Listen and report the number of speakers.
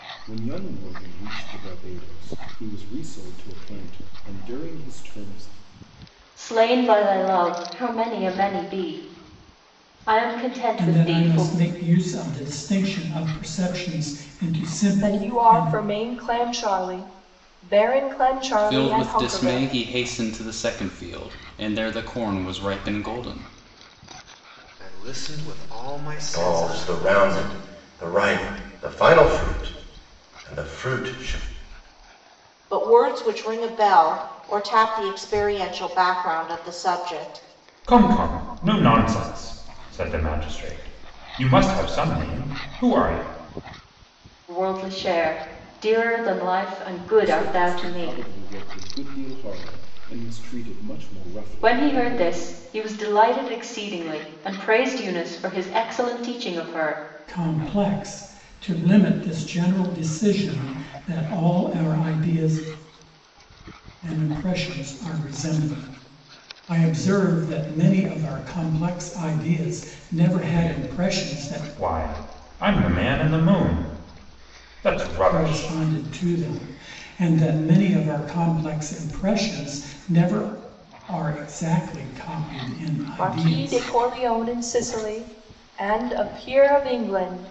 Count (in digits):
9